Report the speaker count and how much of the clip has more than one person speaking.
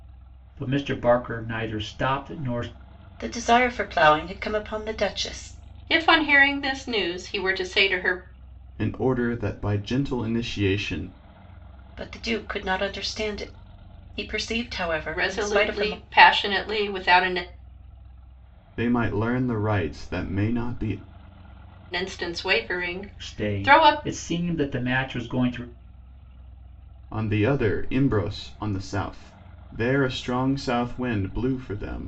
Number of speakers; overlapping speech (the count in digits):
4, about 5%